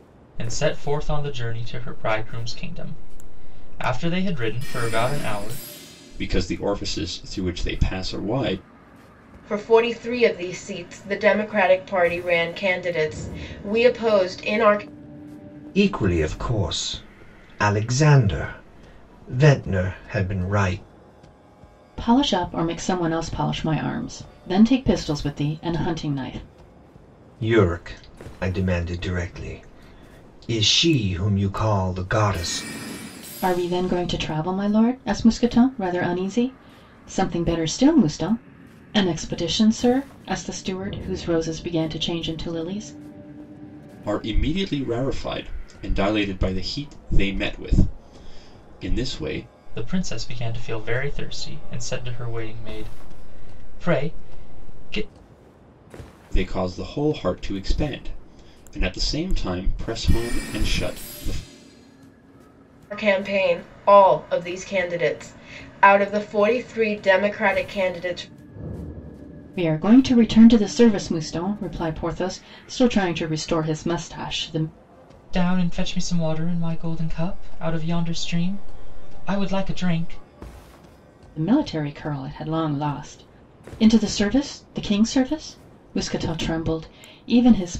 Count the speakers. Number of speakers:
five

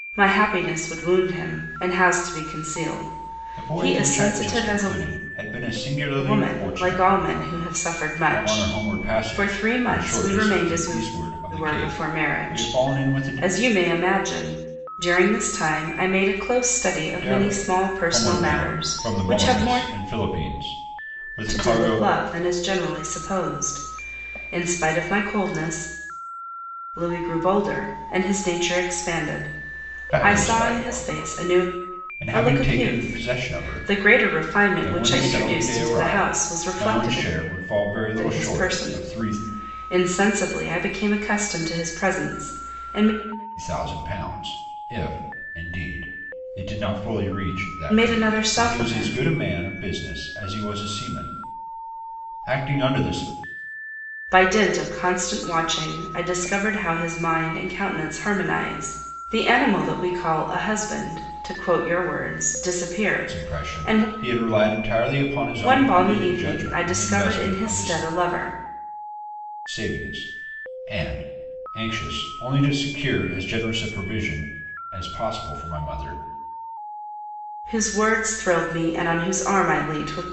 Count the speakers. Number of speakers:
two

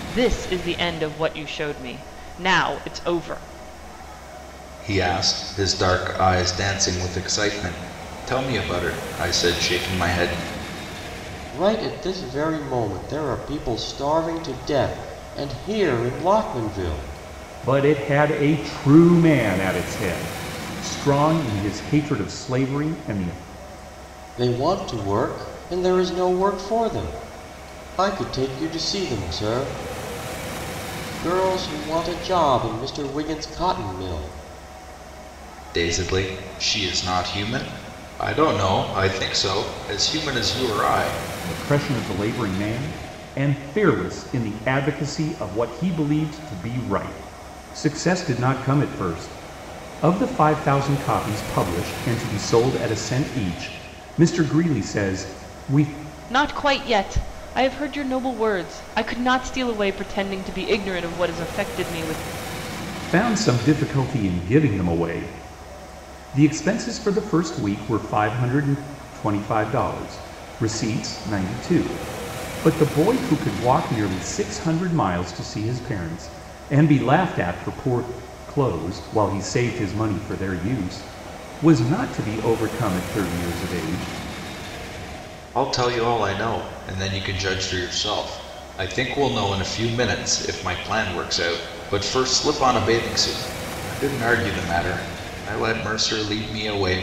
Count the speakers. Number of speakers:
four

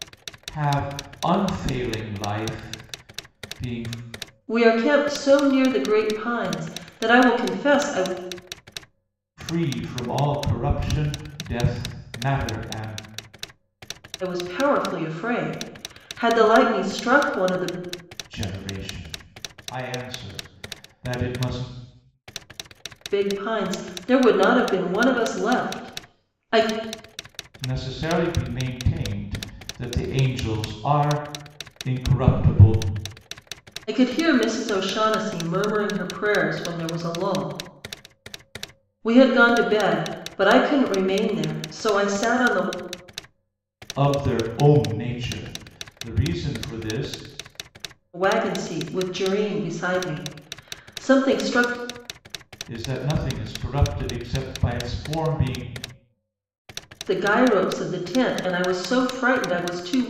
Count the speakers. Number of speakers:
two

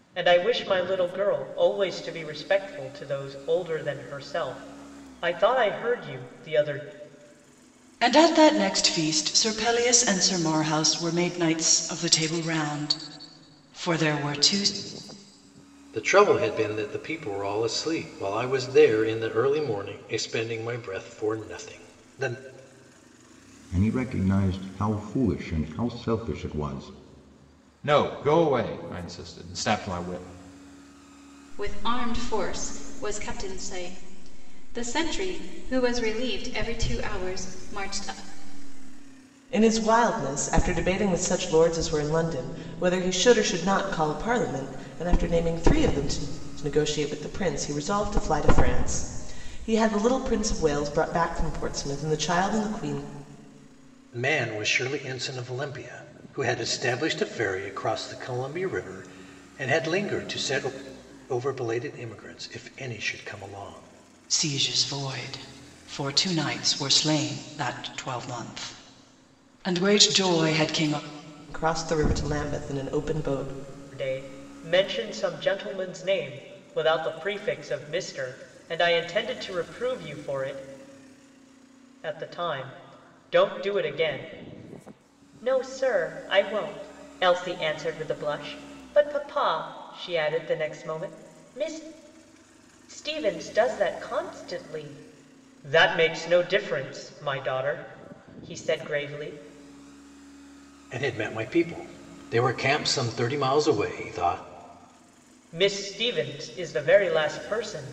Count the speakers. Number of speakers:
seven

